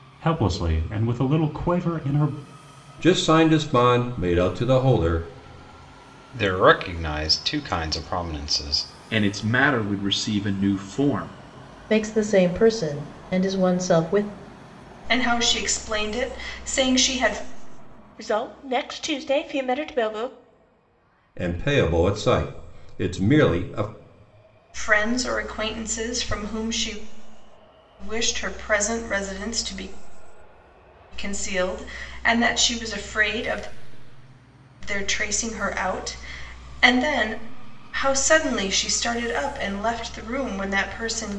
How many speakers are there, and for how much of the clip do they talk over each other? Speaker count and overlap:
7, no overlap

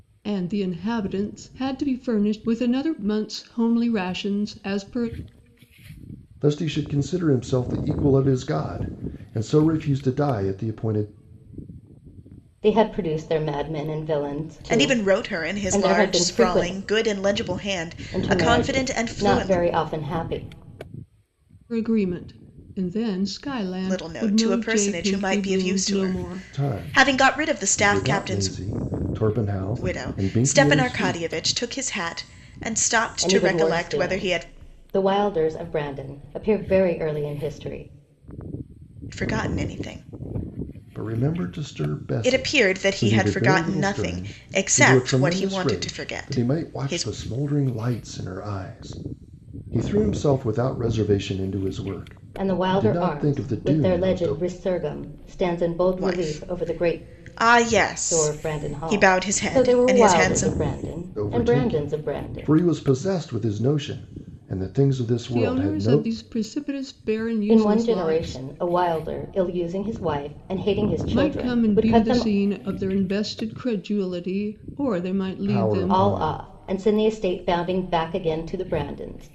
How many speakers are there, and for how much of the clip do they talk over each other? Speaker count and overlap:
4, about 34%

